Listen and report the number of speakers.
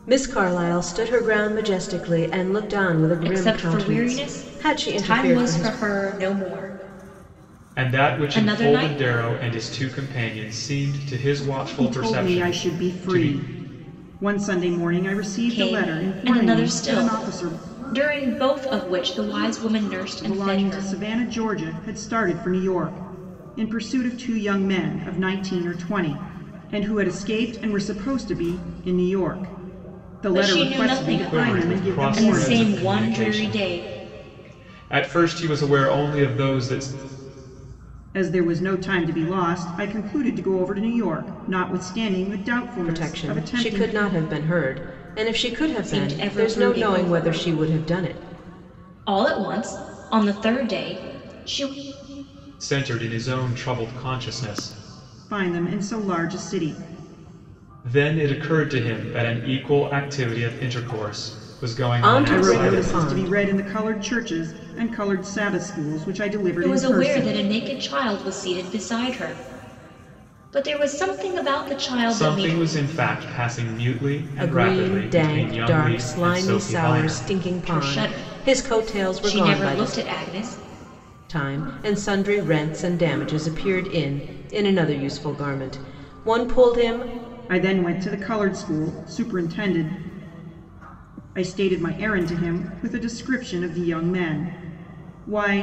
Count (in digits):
4